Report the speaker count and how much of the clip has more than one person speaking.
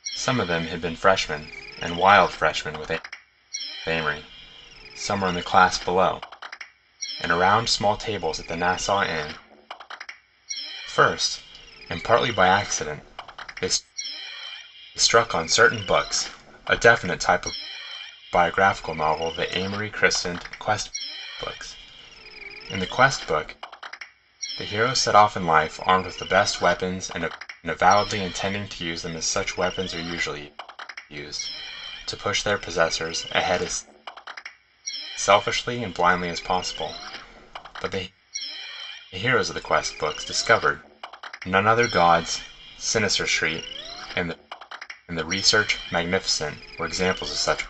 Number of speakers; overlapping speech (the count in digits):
1, no overlap